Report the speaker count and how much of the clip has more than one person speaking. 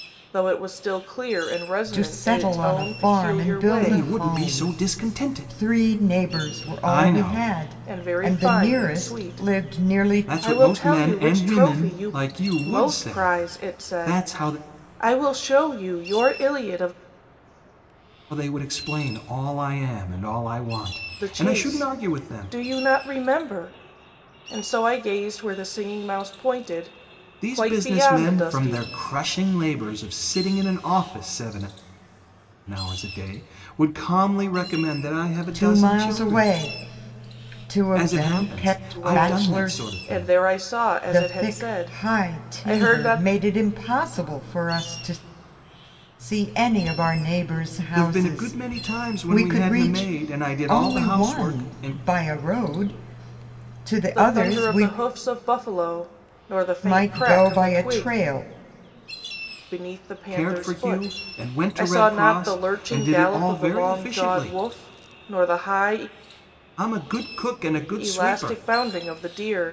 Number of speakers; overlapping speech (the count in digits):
3, about 44%